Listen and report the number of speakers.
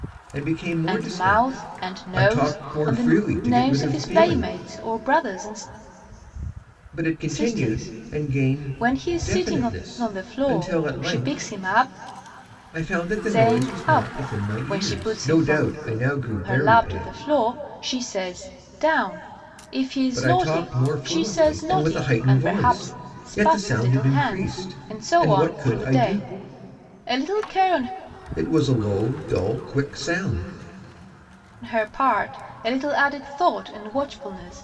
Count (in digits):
2